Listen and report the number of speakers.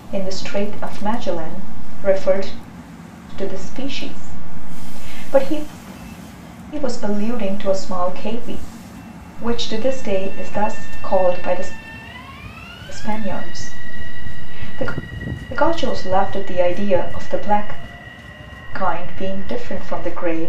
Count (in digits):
1